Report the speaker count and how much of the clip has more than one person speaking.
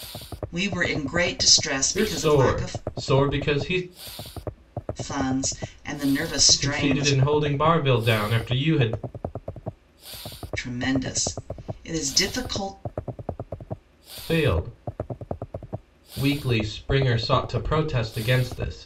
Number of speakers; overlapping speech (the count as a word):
two, about 8%